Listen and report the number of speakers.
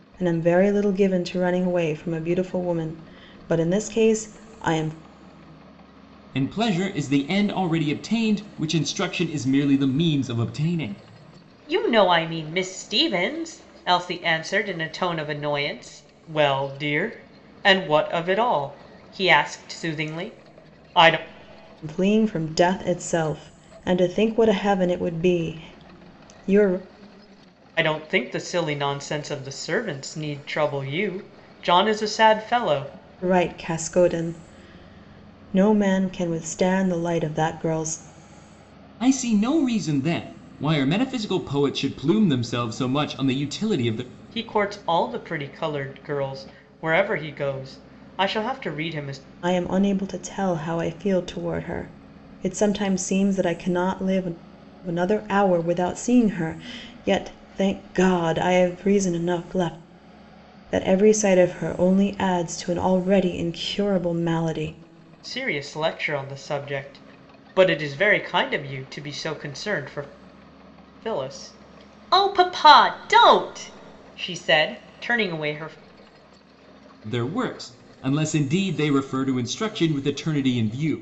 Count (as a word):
three